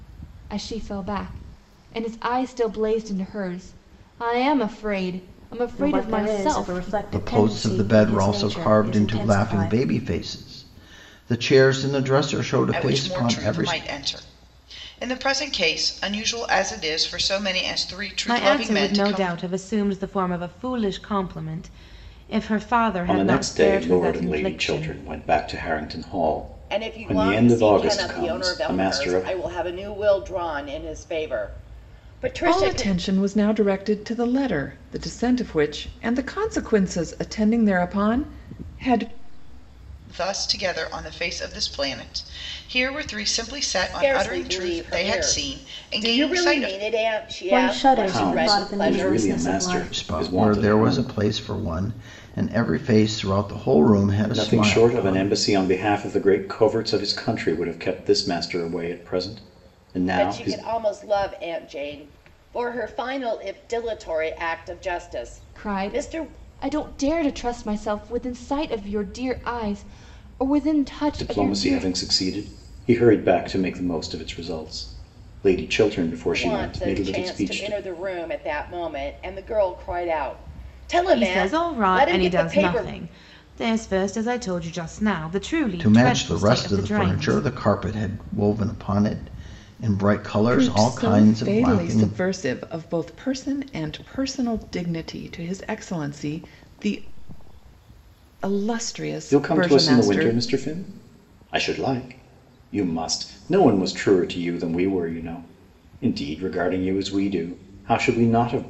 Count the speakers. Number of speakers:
8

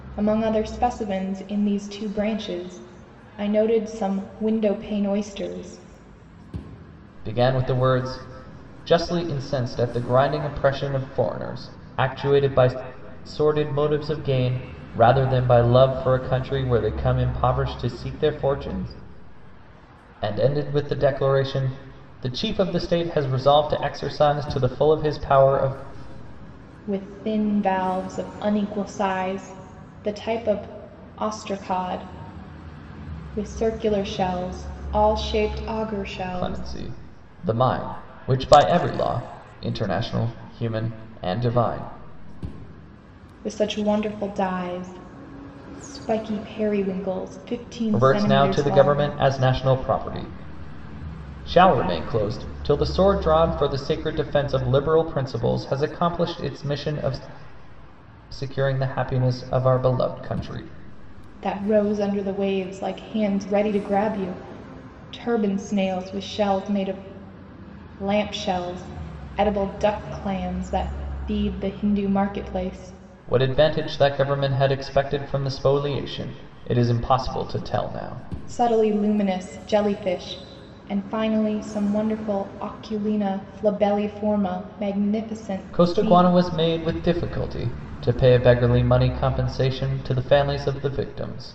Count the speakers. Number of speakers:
2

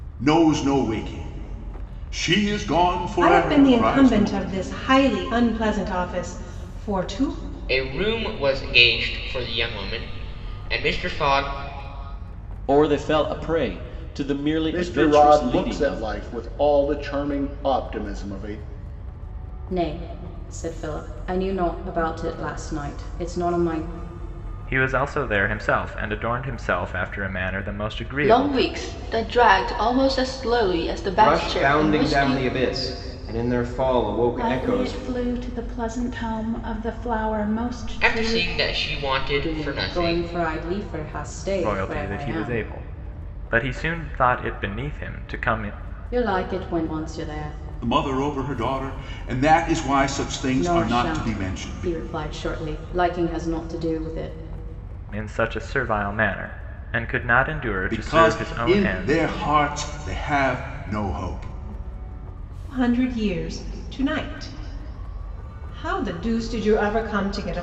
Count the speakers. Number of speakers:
10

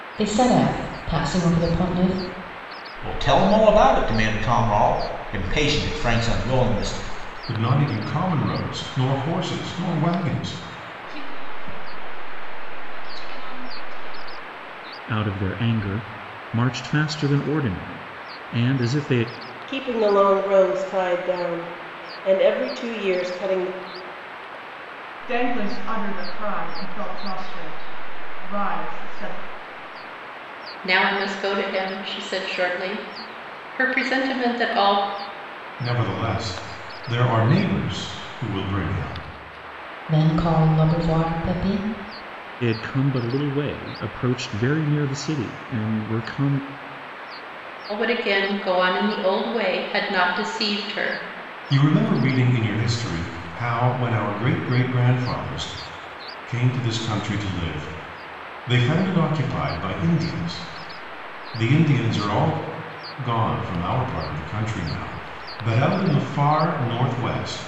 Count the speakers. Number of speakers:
8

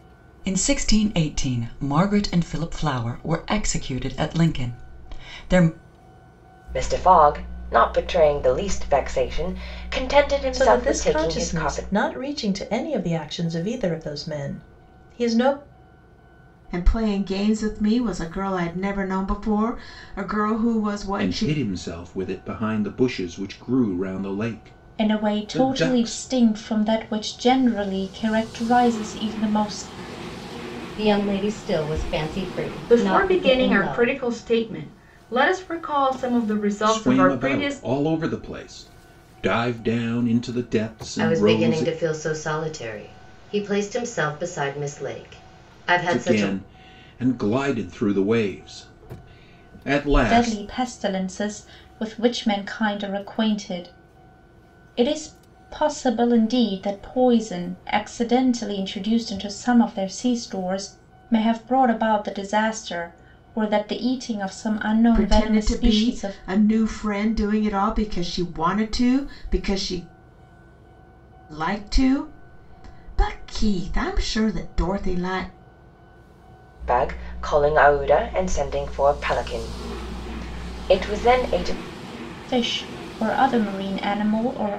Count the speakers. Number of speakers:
8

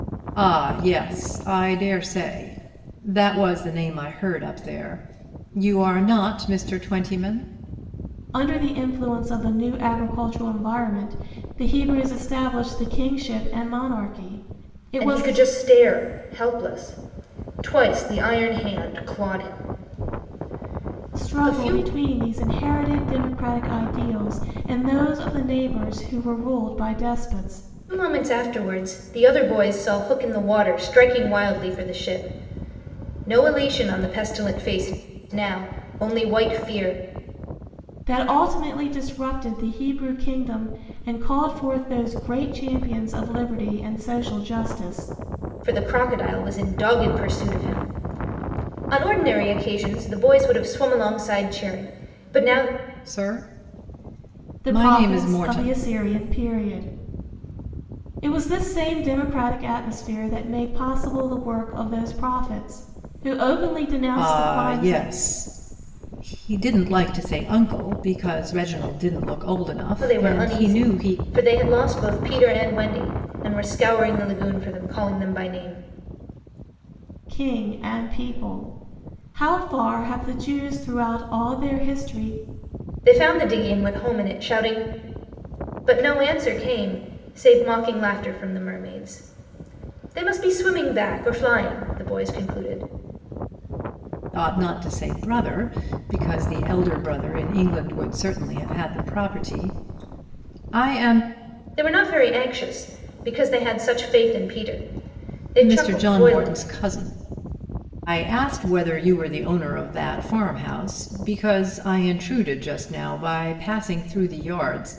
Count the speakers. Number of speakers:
3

